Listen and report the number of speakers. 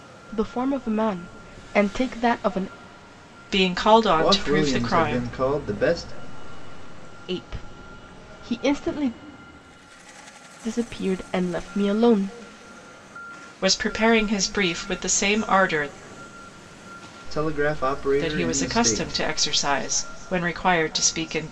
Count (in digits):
3